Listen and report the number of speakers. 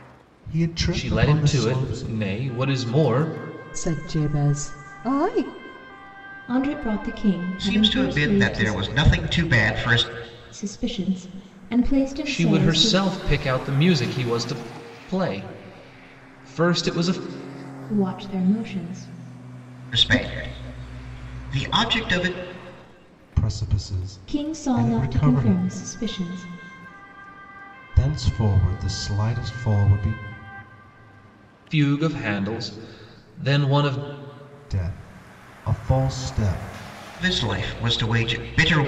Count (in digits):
5